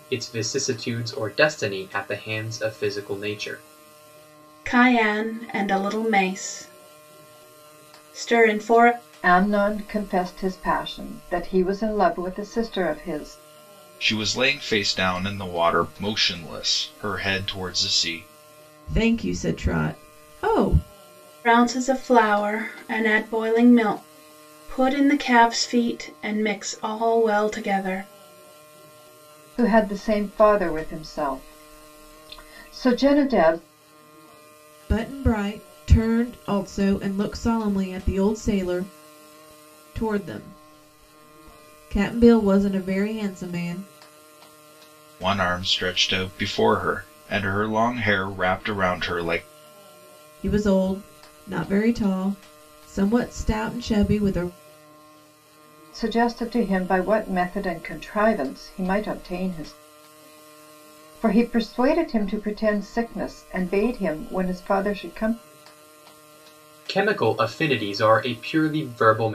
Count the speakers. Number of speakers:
5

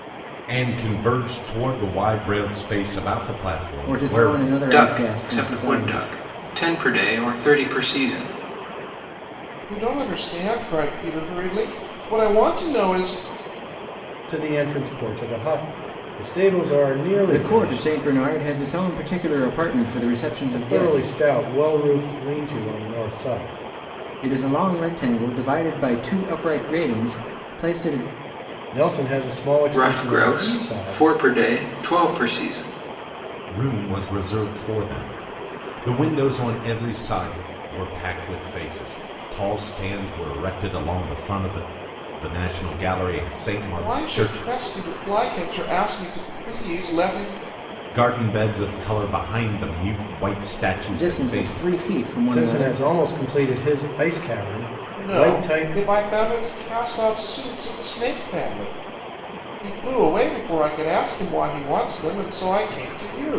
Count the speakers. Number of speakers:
5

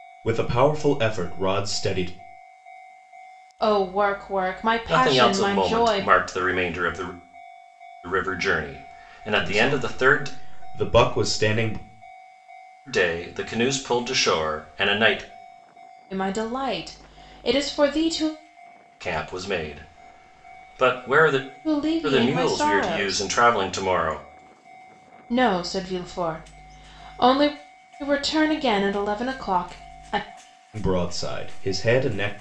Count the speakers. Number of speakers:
3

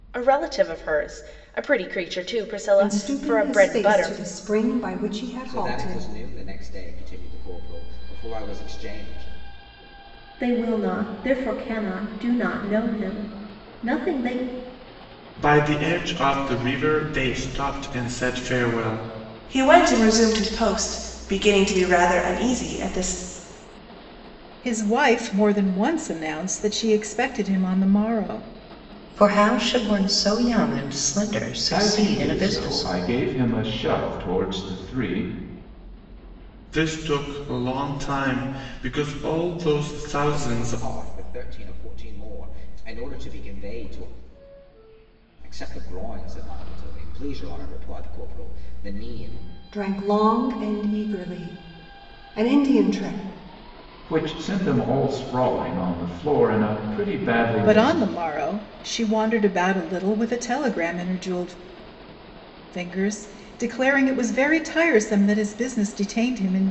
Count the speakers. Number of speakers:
9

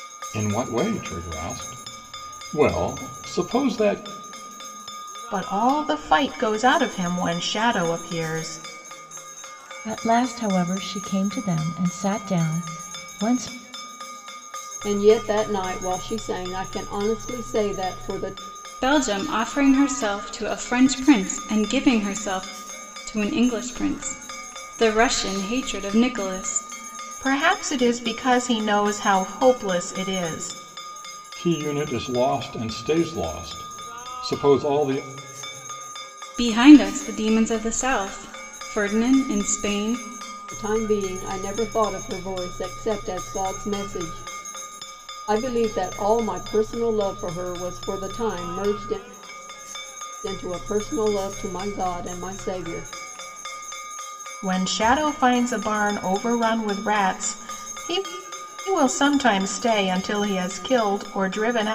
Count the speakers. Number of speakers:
5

